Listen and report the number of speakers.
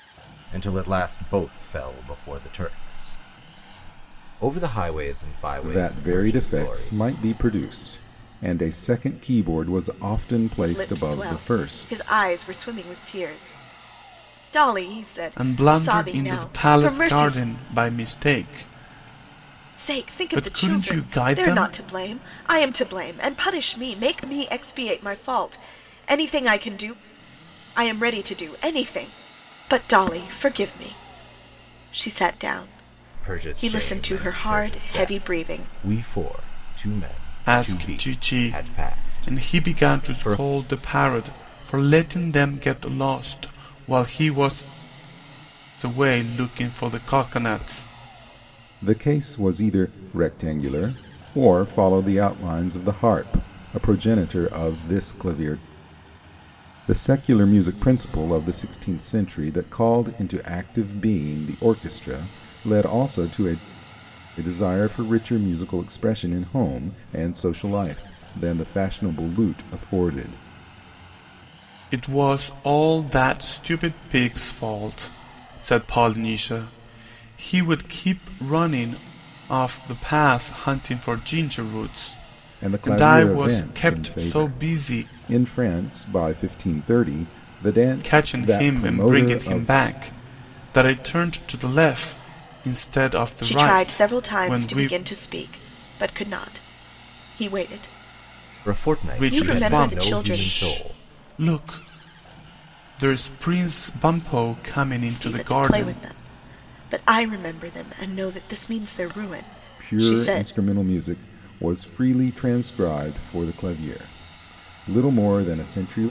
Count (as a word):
four